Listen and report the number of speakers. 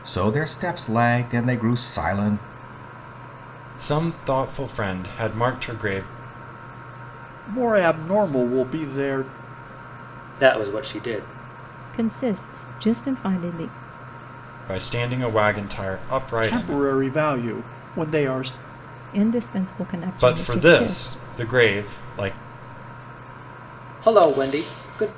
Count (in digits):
5